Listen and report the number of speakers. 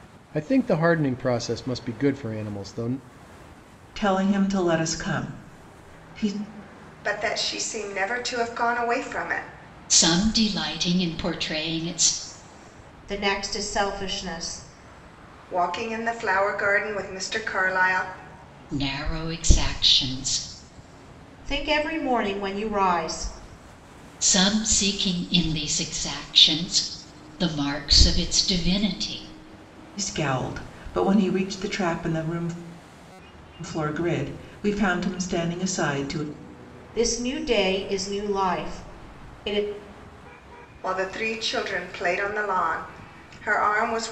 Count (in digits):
5